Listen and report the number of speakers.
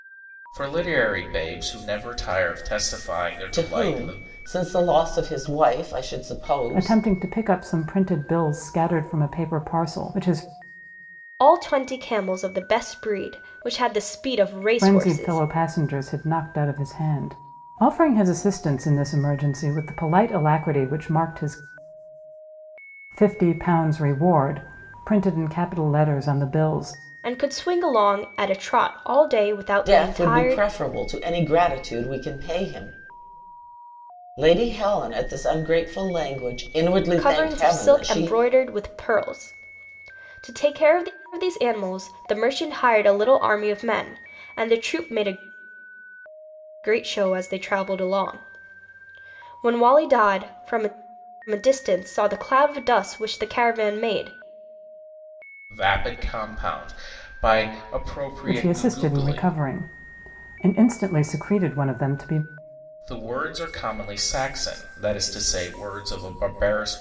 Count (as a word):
four